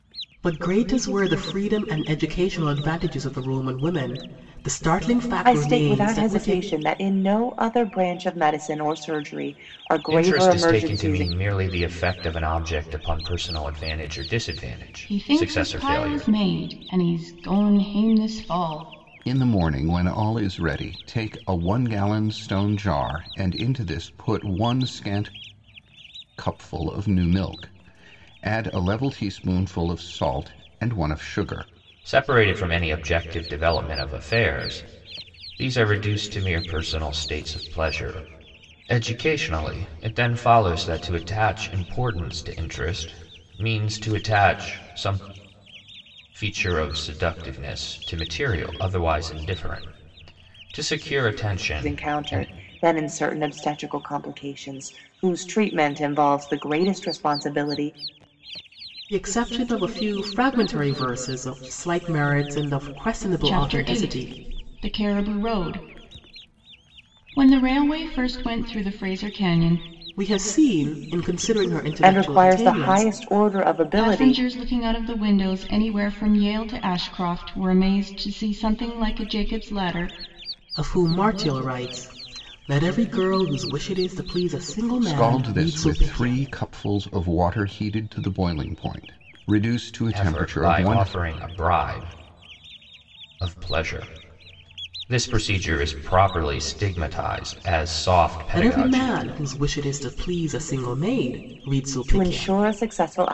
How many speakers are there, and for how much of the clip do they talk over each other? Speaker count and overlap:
5, about 10%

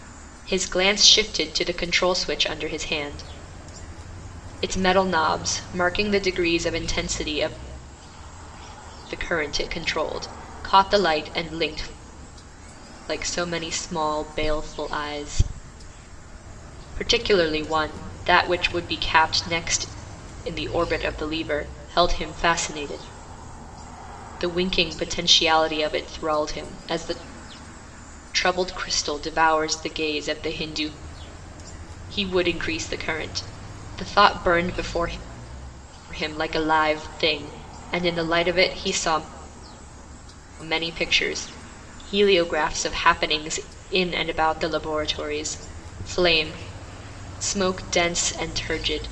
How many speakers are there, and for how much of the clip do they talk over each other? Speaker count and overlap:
1, no overlap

